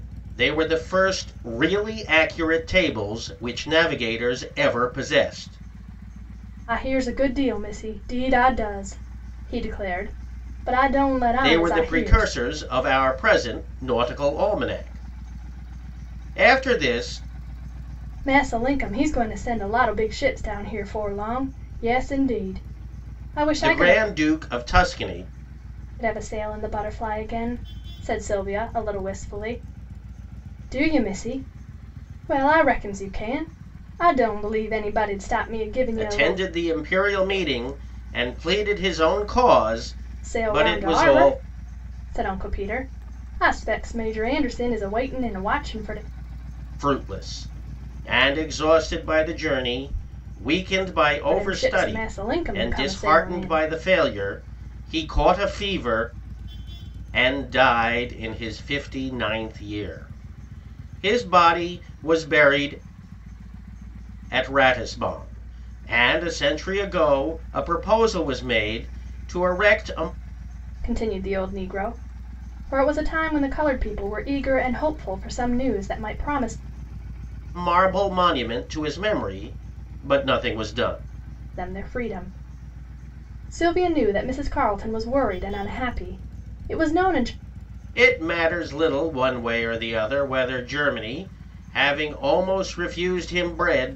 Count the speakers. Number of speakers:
2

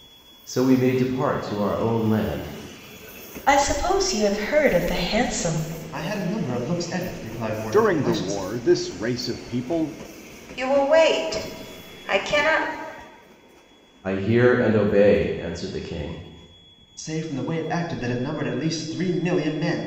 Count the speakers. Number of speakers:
5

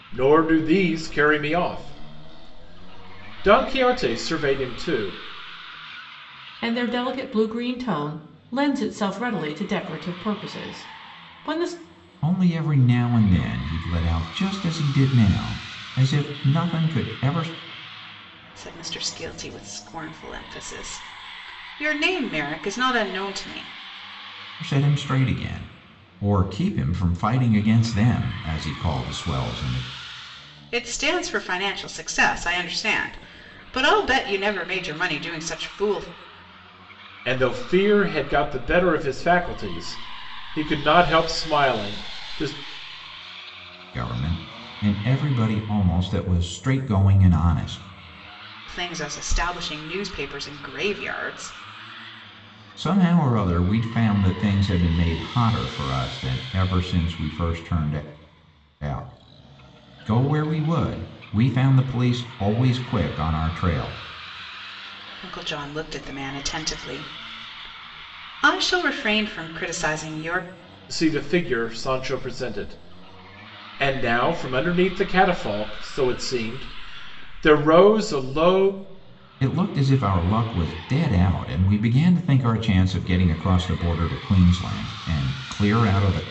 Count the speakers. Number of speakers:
4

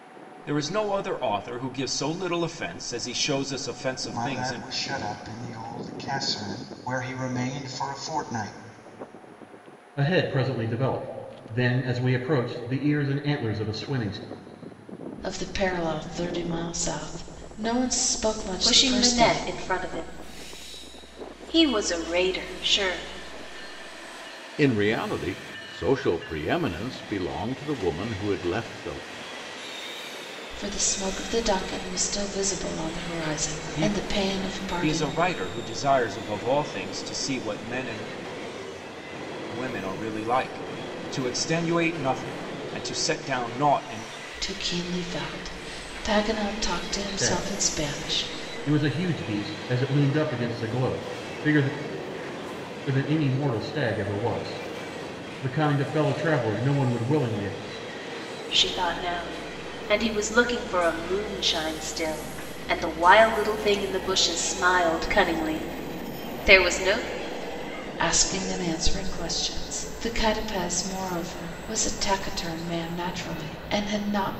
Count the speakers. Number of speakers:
6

